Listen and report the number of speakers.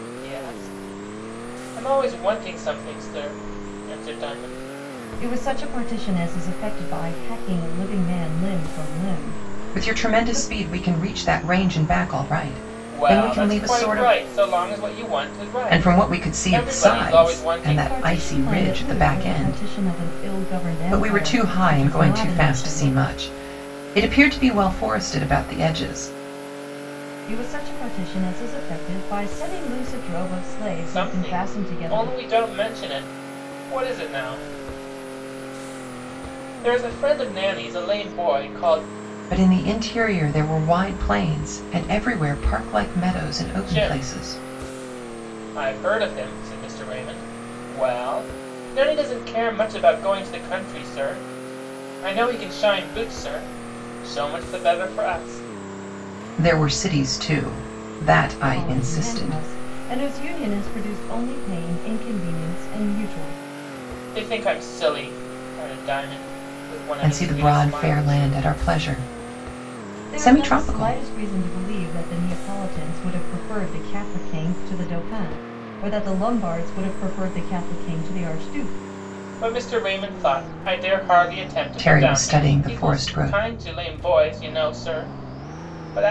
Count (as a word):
three